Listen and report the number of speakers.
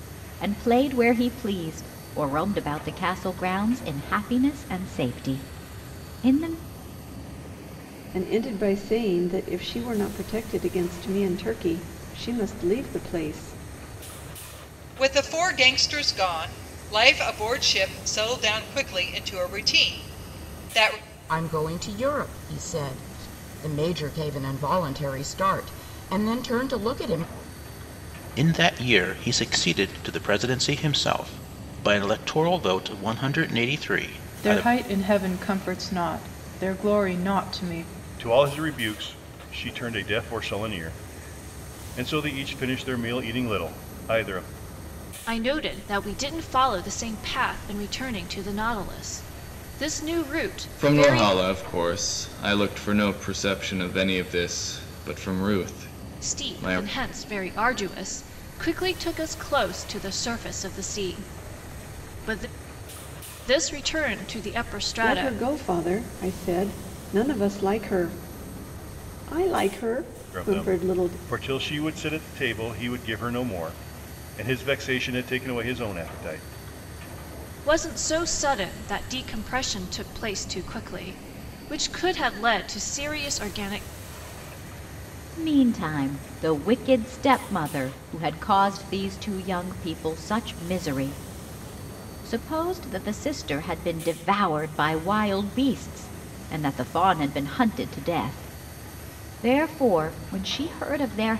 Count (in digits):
9